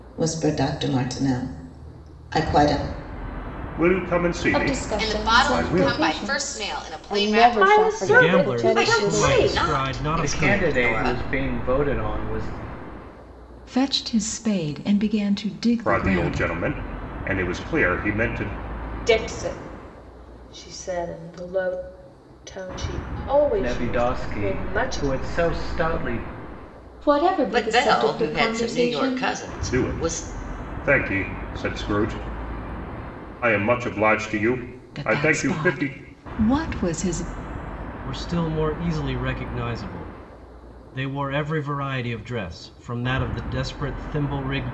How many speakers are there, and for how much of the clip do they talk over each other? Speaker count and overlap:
10, about 27%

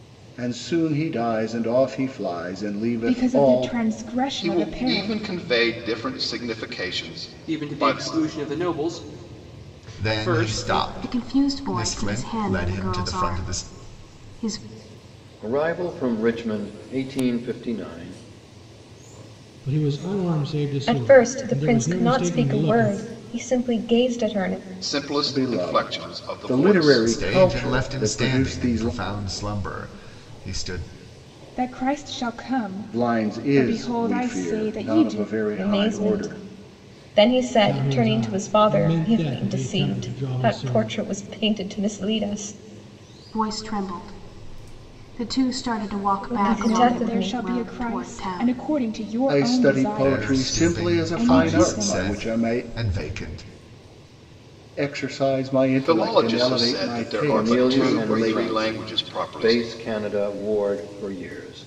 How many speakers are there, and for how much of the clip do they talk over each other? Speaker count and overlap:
9, about 45%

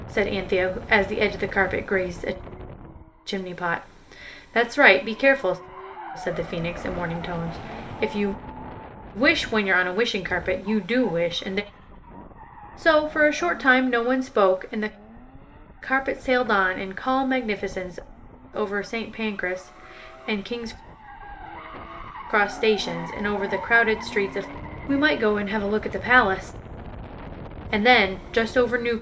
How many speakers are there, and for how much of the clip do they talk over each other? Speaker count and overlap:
1, no overlap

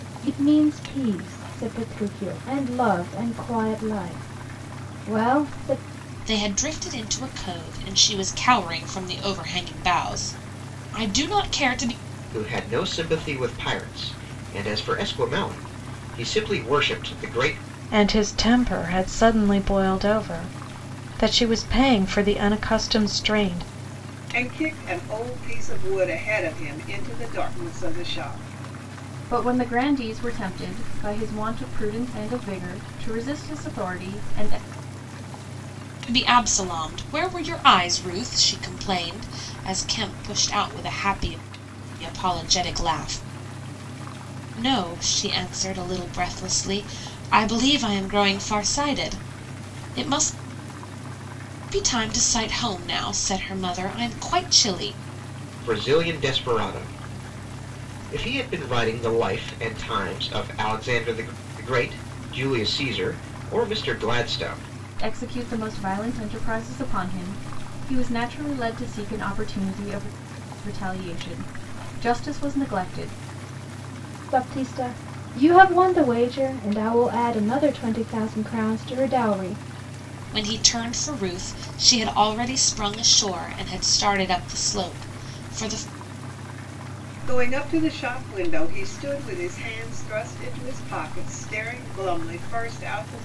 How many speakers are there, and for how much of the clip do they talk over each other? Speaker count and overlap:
6, no overlap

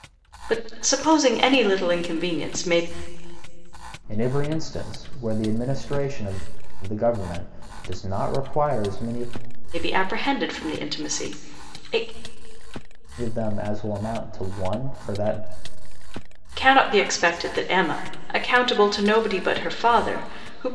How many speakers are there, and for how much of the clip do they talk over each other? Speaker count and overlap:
2, no overlap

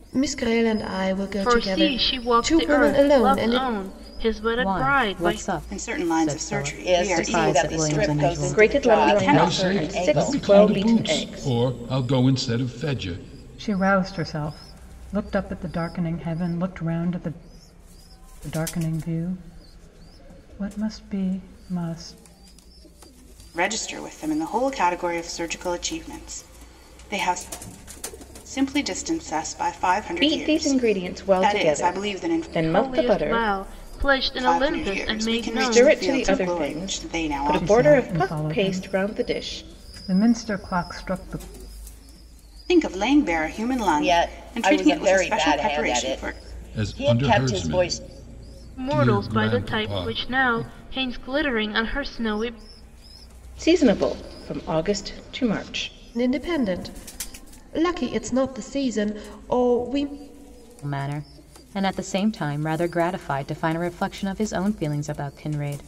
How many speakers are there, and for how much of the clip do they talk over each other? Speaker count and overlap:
8, about 35%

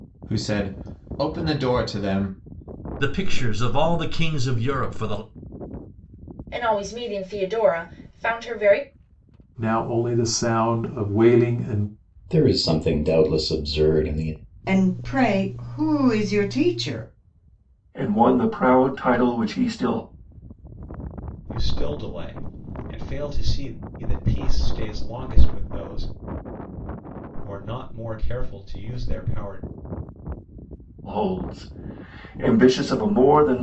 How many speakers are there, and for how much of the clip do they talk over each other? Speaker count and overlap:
8, no overlap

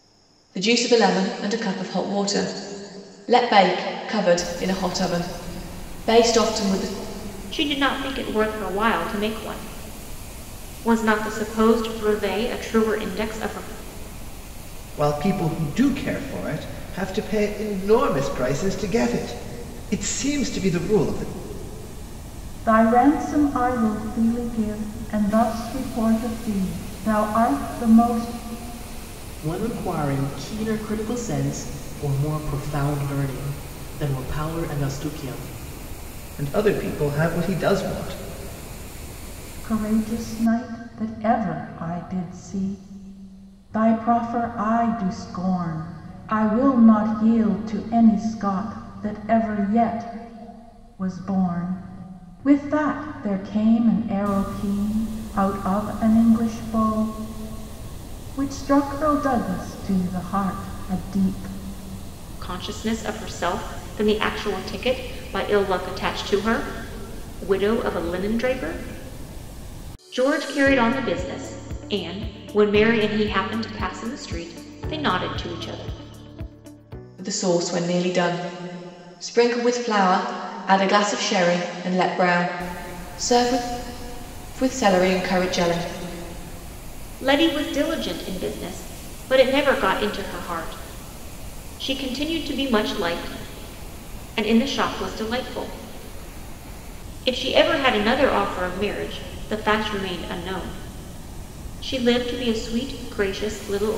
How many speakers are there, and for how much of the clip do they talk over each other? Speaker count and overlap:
5, no overlap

